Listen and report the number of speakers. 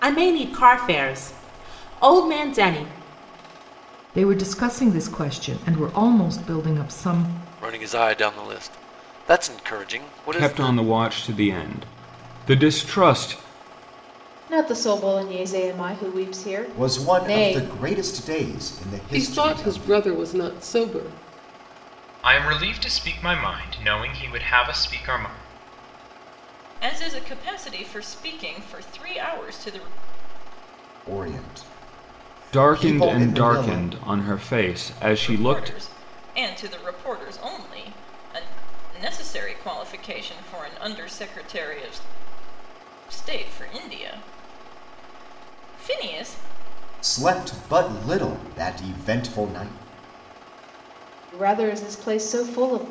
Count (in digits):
9